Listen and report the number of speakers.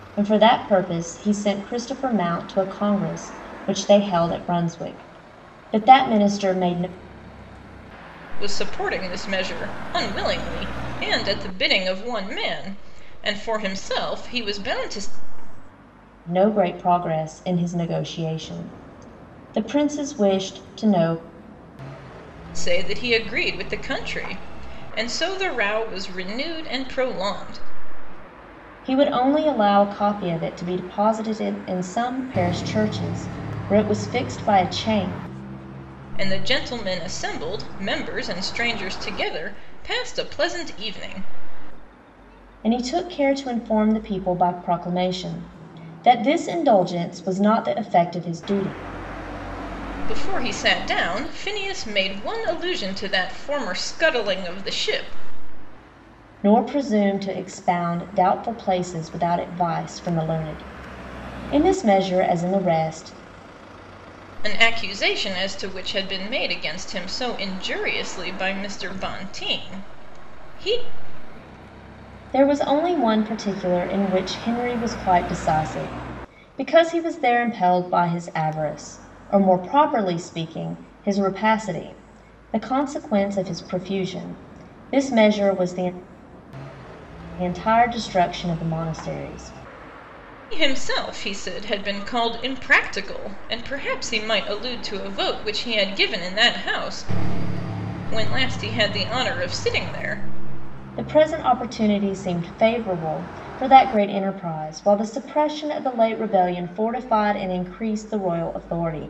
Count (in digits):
2